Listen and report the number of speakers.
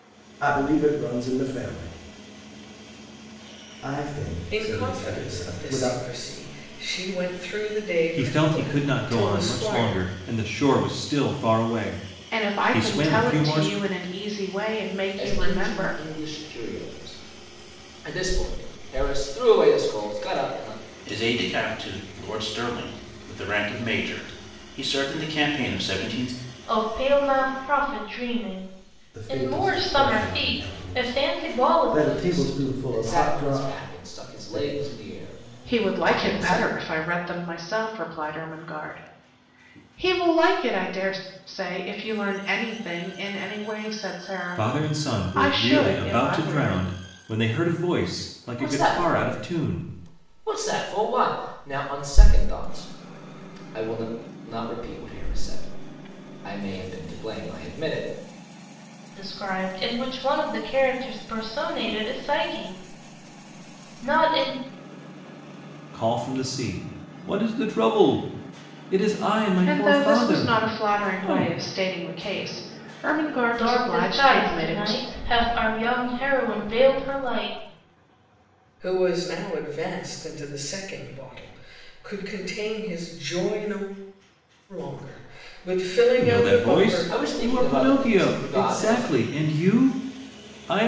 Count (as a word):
seven